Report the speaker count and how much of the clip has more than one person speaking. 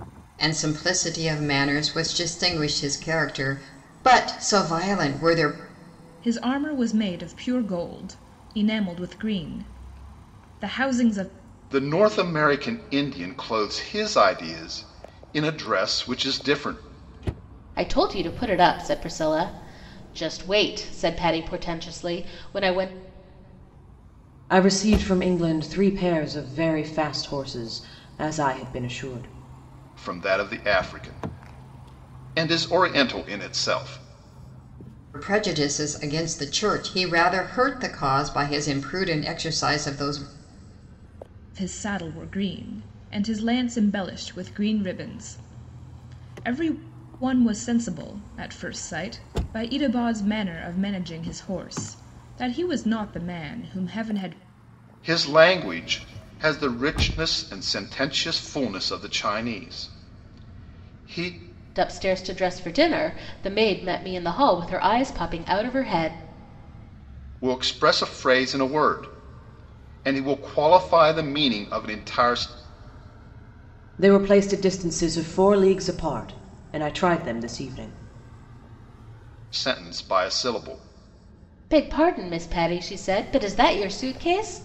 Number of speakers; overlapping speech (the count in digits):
5, no overlap